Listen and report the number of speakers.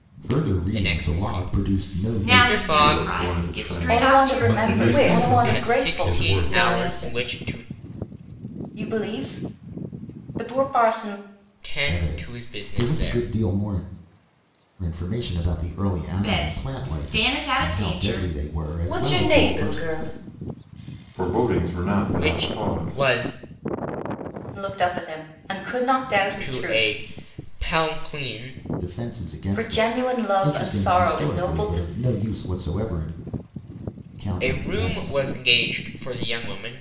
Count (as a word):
seven